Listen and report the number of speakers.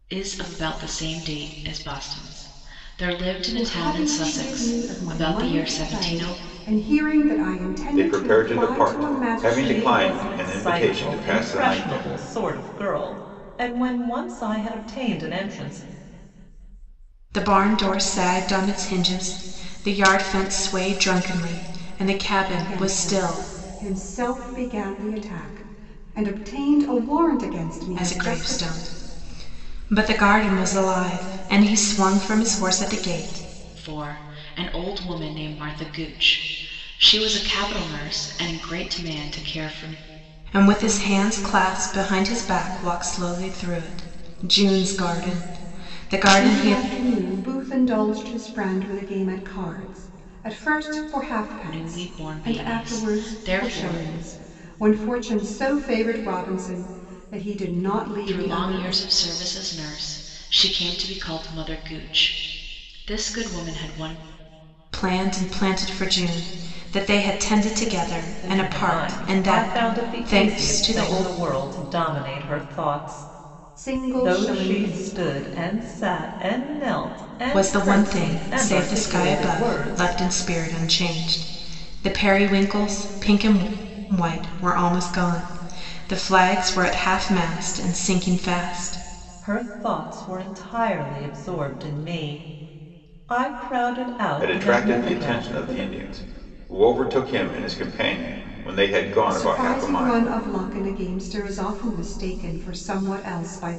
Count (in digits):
5